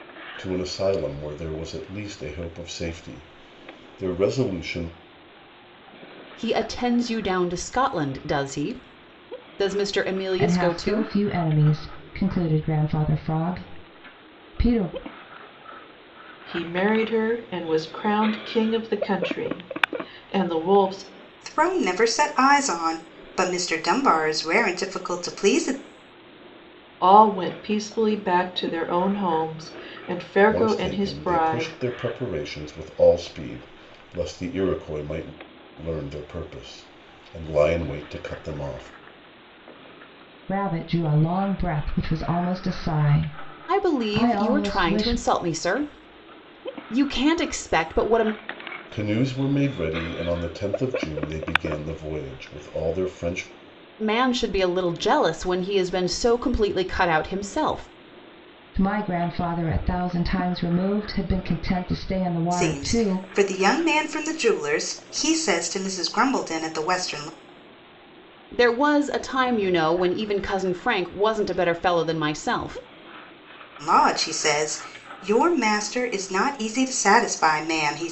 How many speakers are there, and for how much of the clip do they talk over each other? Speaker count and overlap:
5, about 5%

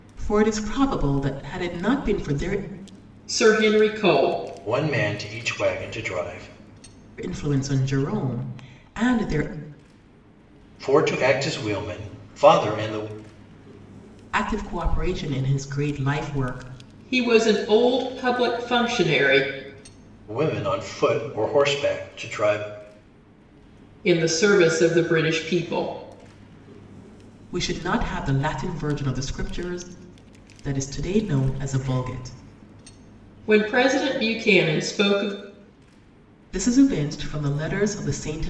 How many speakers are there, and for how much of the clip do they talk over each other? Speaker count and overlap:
3, no overlap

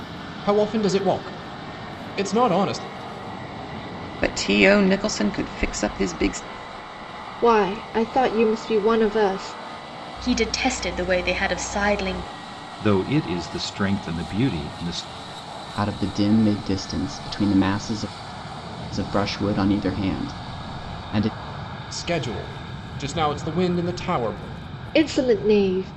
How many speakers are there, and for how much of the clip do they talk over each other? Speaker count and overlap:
6, no overlap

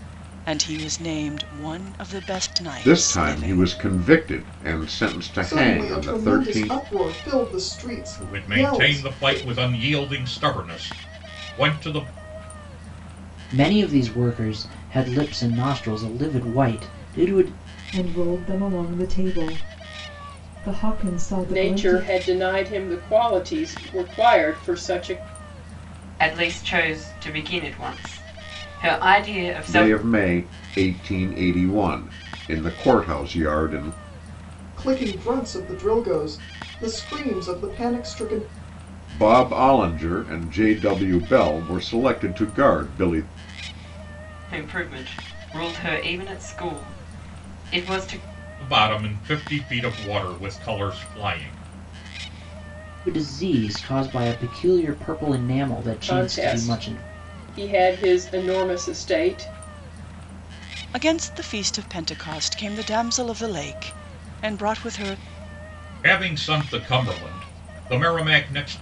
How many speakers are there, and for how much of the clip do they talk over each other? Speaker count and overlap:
8, about 9%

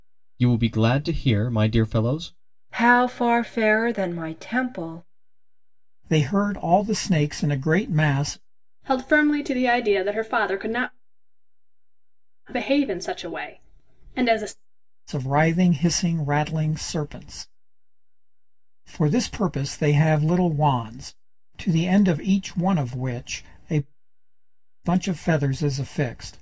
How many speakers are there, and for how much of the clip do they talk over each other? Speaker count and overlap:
4, no overlap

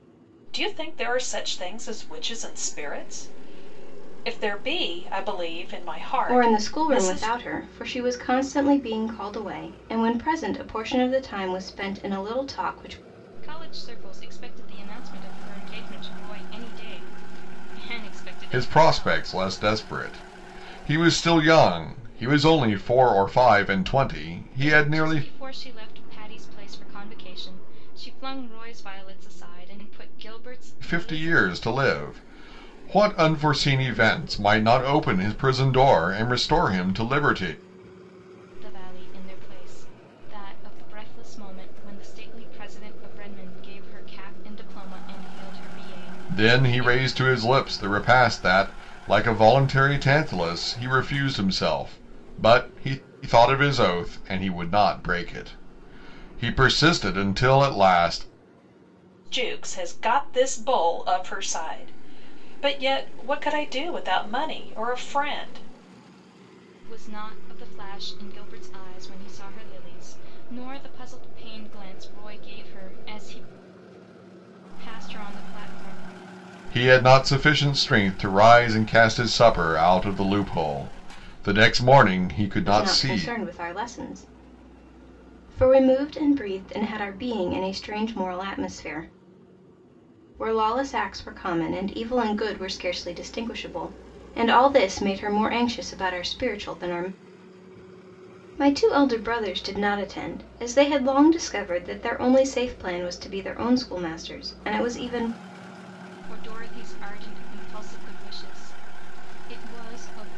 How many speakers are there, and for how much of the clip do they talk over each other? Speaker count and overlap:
4, about 4%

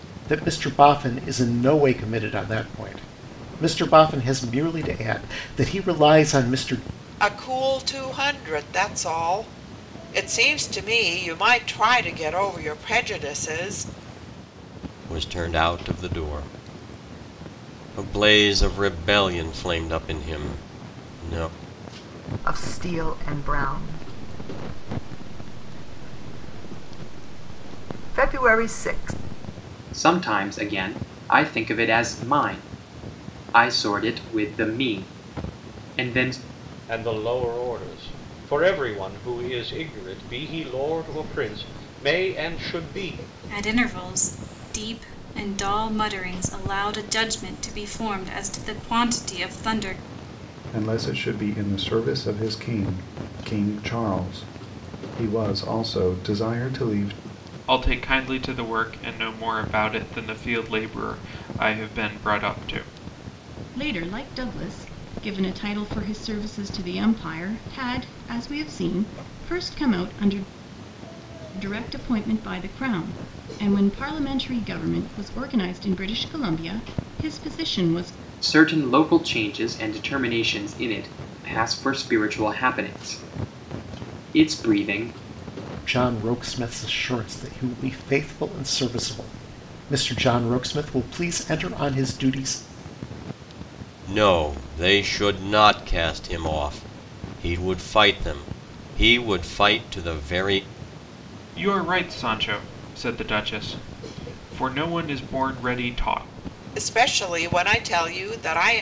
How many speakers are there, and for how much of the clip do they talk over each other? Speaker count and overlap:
10, no overlap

